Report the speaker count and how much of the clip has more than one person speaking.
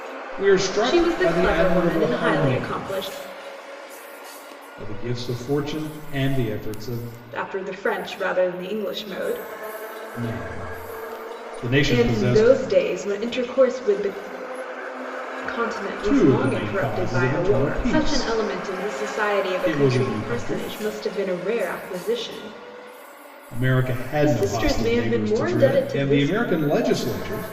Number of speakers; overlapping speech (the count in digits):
2, about 30%